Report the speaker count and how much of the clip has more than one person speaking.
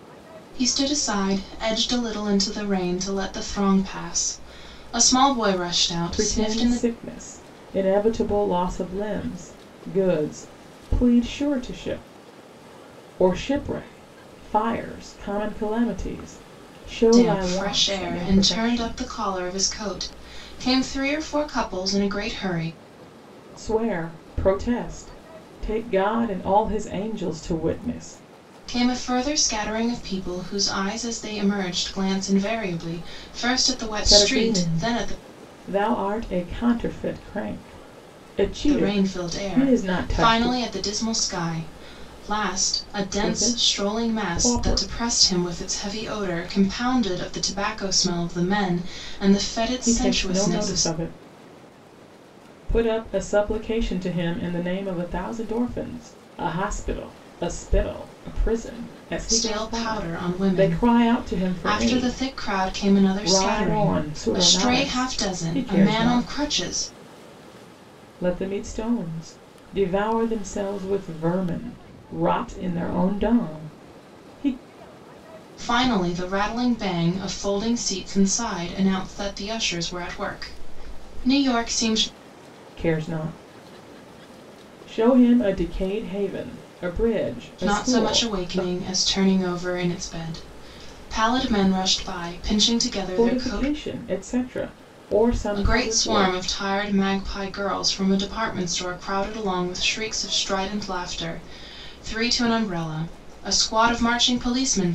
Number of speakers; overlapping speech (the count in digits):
2, about 17%